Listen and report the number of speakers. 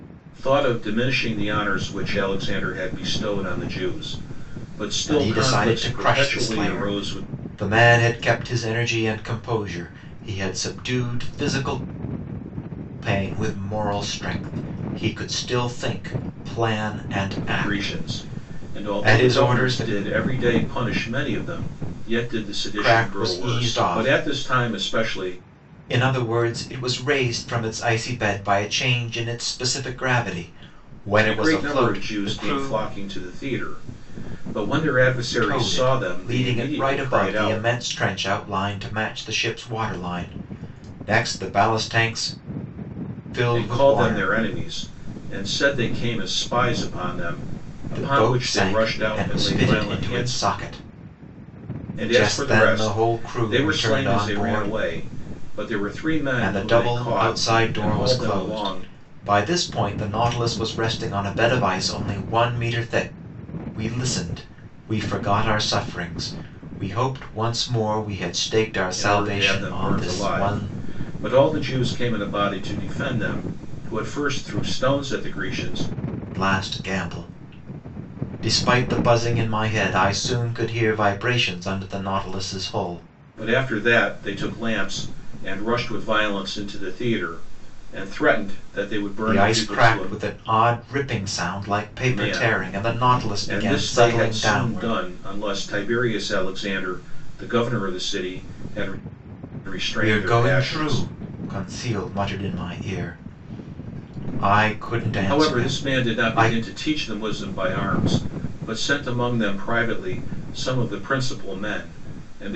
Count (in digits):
2